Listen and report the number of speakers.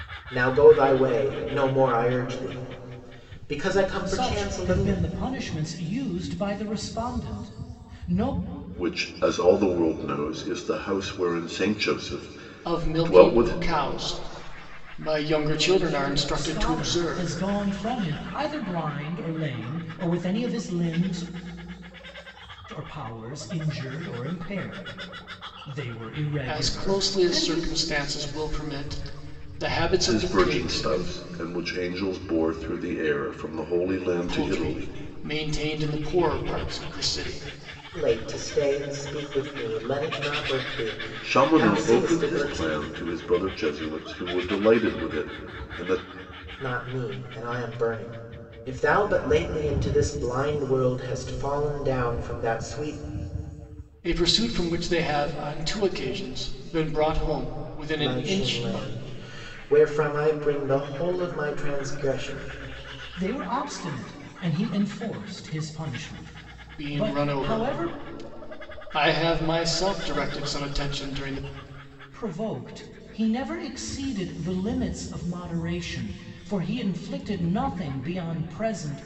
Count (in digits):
4